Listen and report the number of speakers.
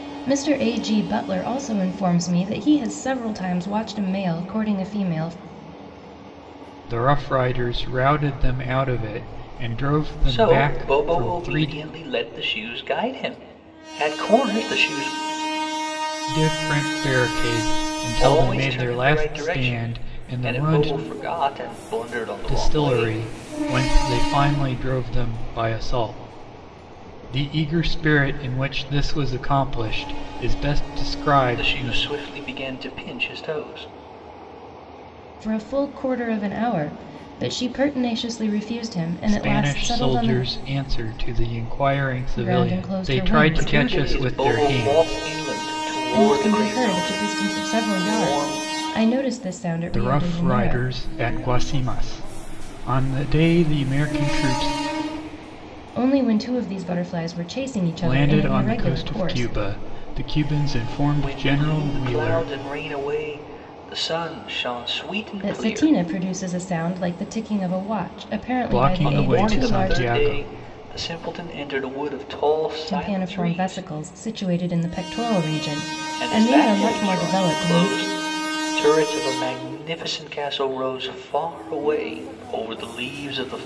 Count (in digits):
3